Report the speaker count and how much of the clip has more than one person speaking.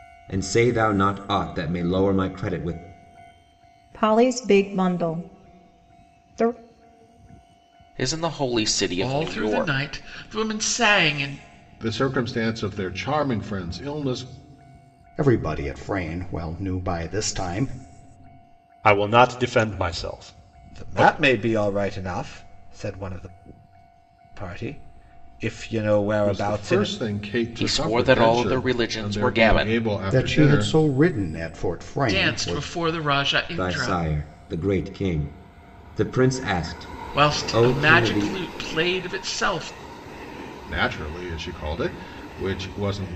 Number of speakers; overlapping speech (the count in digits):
8, about 16%